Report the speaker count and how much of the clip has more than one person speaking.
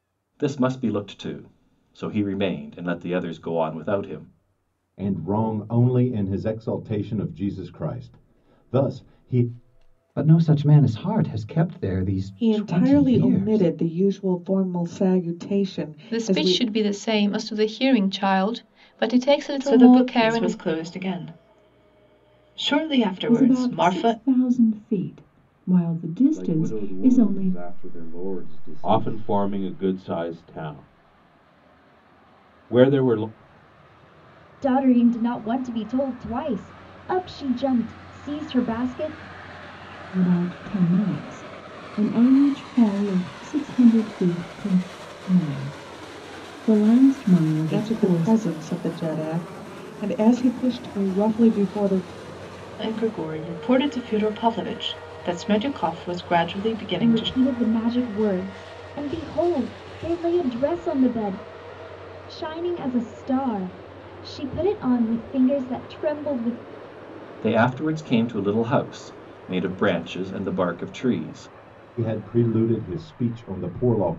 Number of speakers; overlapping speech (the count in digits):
10, about 9%